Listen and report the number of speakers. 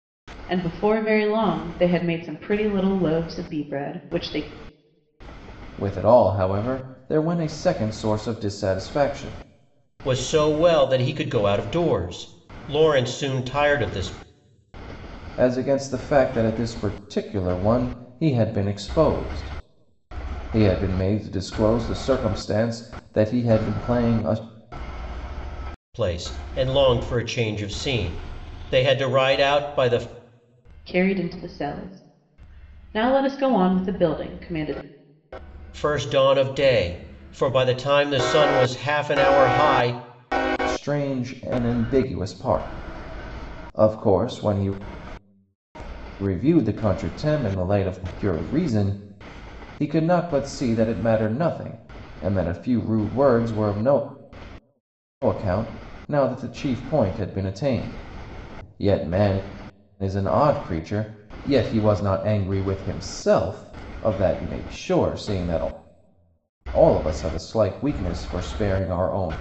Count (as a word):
three